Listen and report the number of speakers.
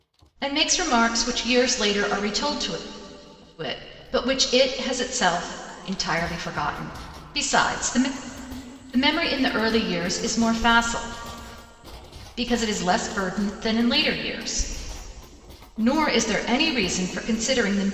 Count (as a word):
one